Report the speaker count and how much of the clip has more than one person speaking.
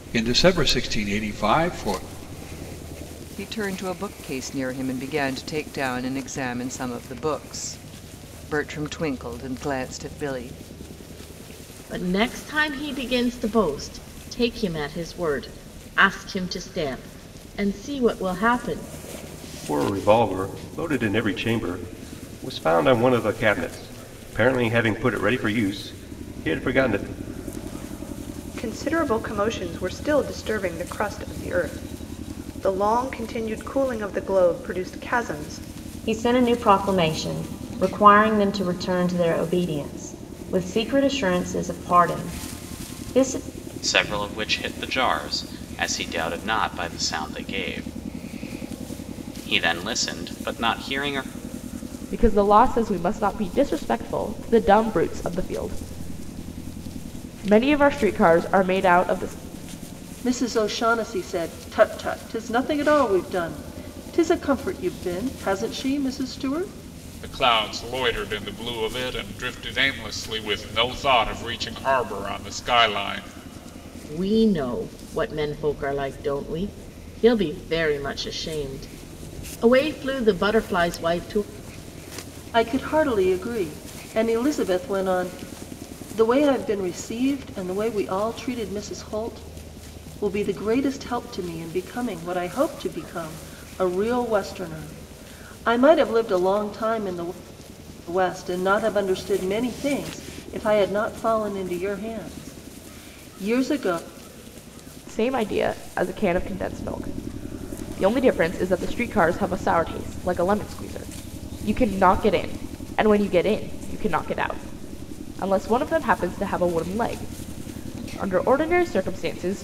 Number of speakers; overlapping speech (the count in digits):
10, no overlap